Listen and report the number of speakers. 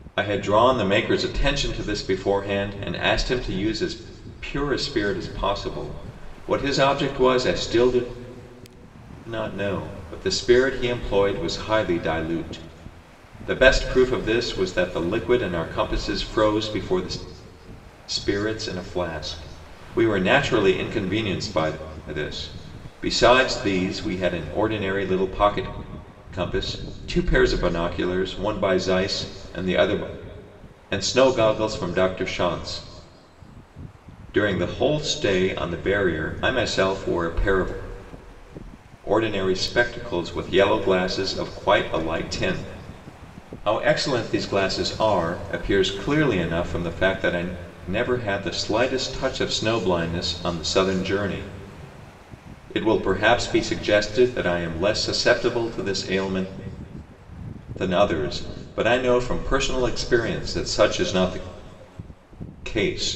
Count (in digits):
1